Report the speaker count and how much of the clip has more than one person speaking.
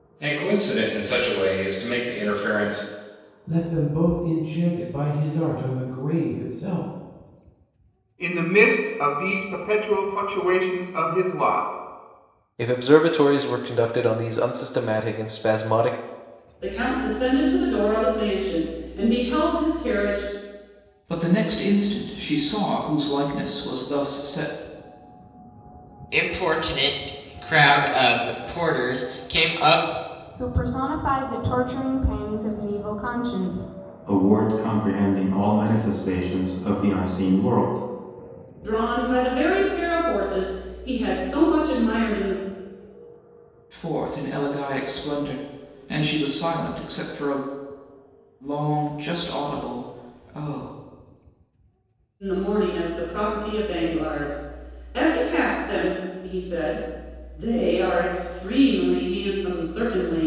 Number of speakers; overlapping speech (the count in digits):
9, no overlap